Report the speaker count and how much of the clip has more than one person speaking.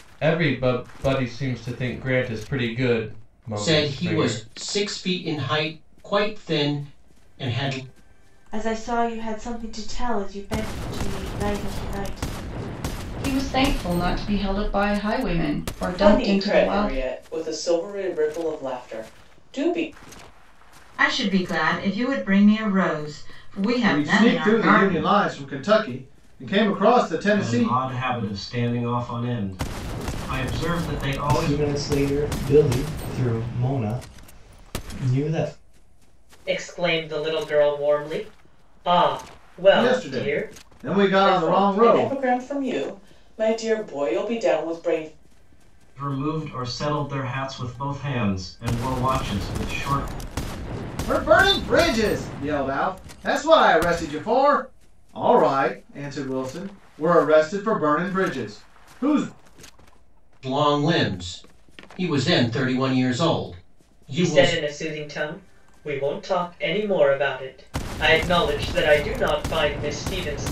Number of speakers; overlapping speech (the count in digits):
10, about 9%